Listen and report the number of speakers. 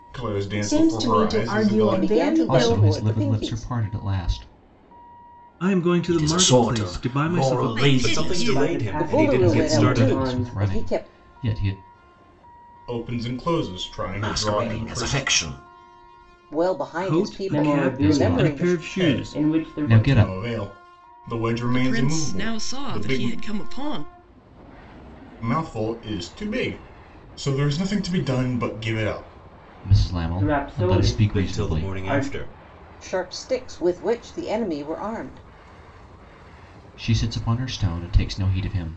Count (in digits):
9